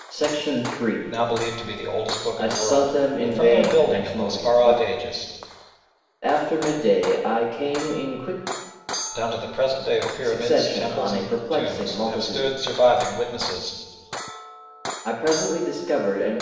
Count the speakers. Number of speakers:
2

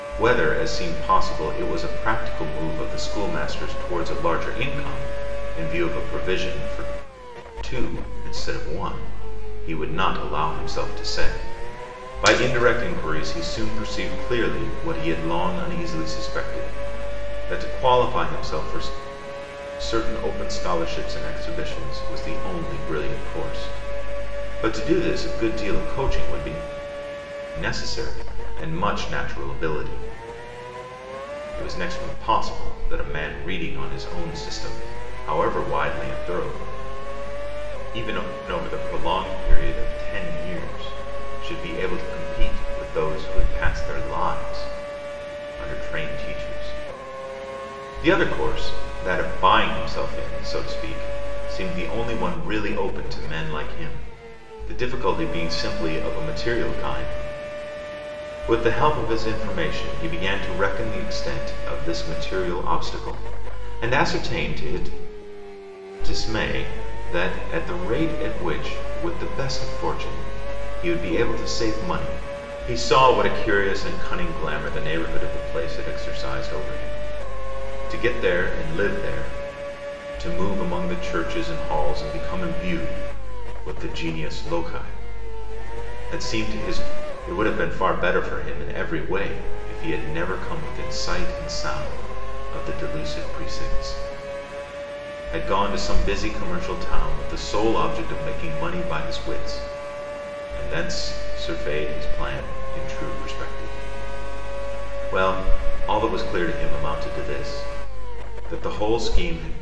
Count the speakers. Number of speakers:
1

